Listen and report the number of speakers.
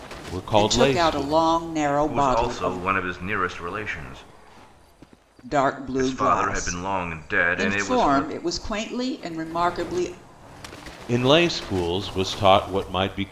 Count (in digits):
3